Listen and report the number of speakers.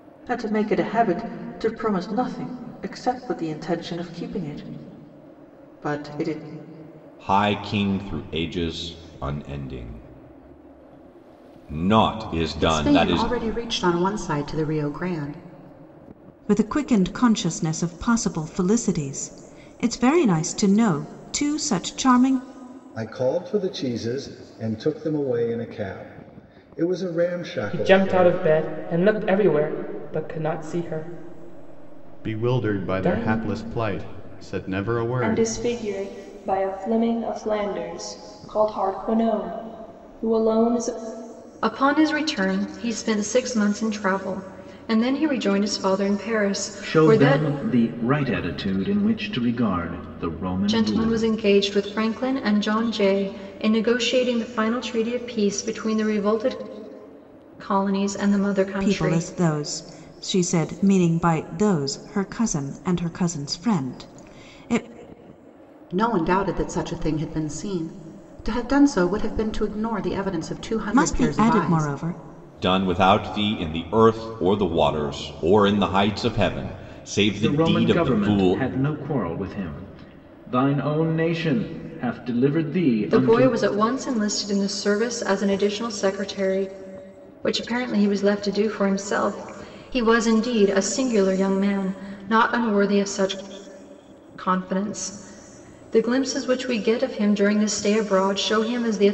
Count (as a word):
ten